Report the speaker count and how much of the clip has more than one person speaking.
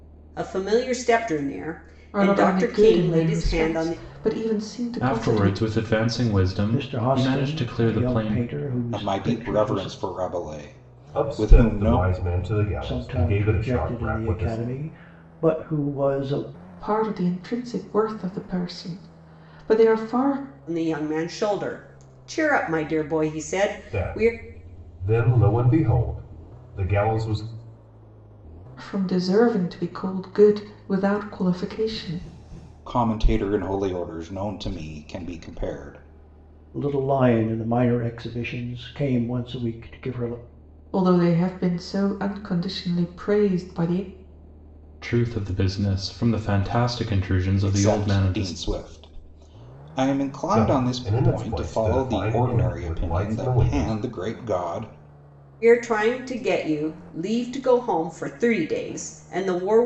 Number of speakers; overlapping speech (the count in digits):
6, about 22%